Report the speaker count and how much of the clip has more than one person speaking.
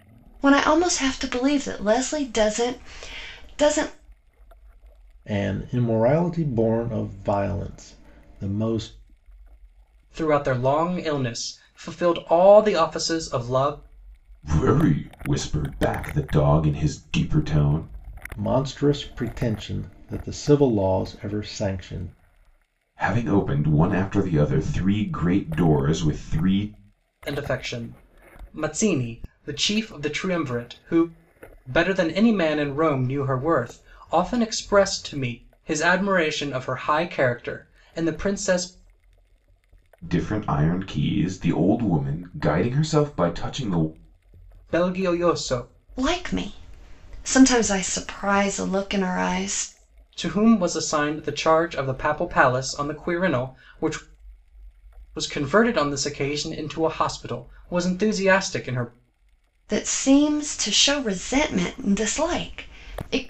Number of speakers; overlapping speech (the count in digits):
4, no overlap